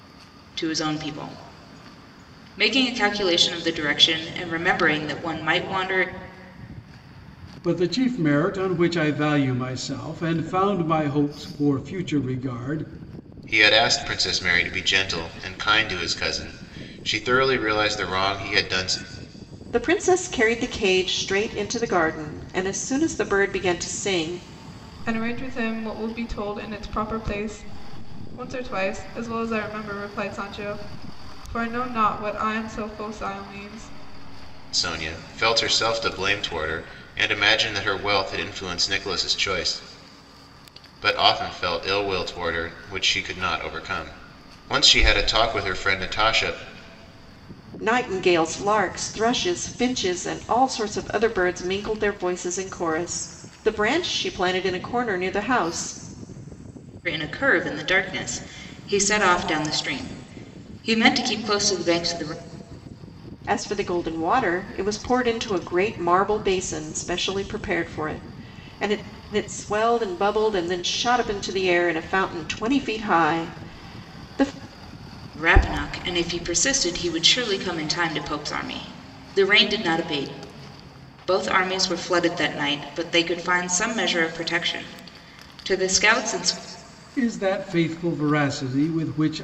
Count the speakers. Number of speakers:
five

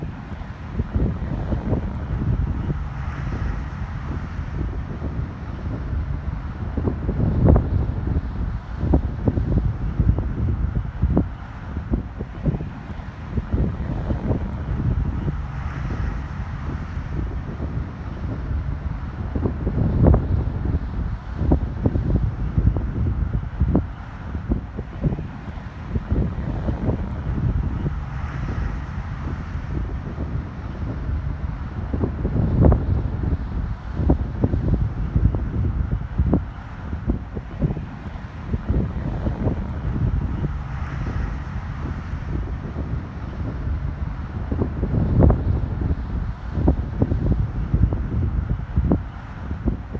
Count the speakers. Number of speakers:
zero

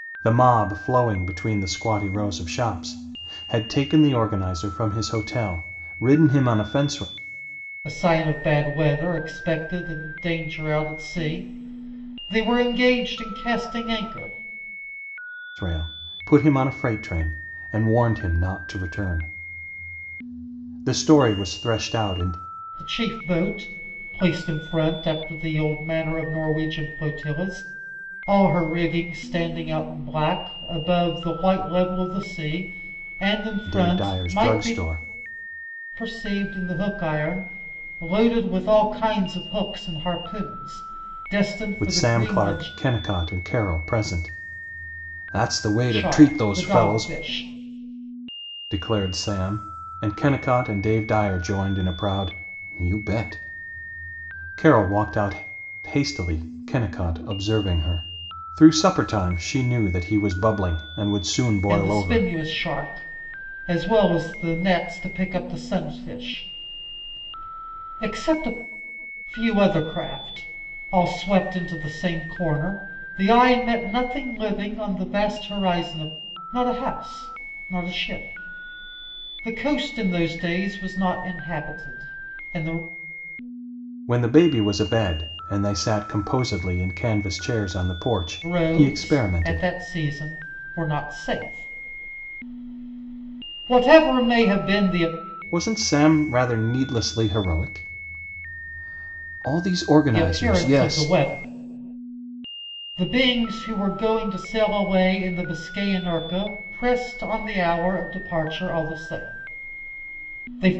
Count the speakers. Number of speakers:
two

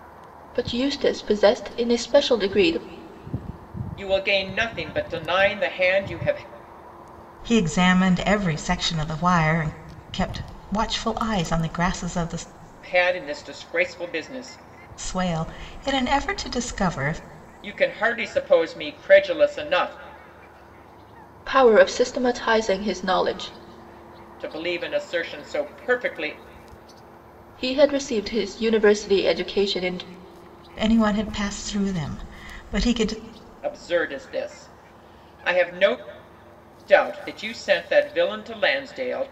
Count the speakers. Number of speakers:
three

